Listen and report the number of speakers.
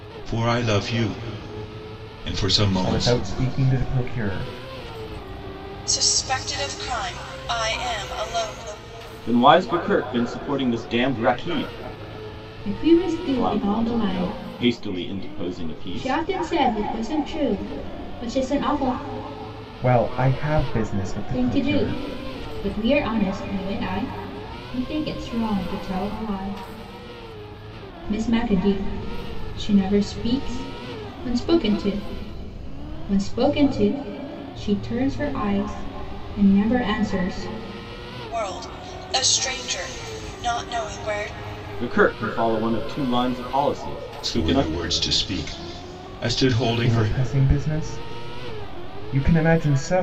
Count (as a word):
five